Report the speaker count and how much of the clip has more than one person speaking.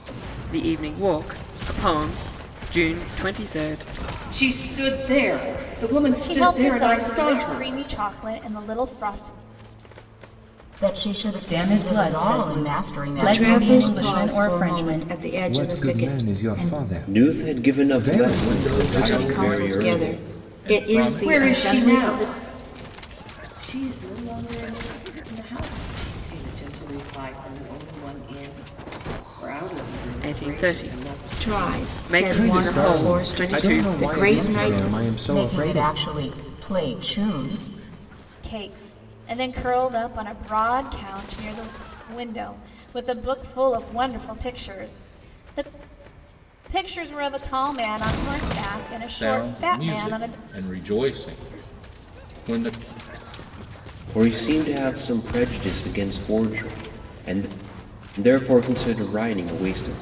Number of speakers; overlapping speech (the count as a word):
nine, about 31%